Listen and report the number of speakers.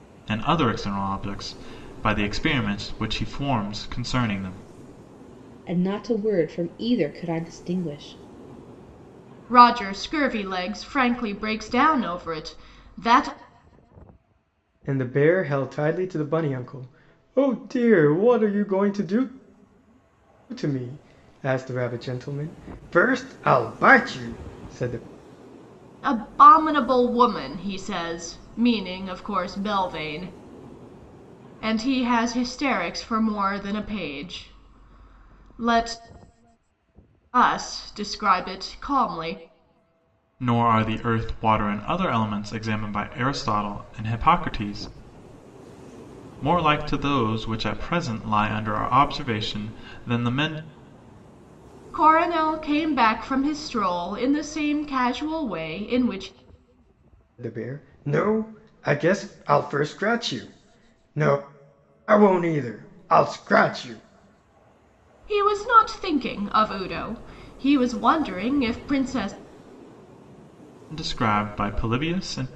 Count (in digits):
4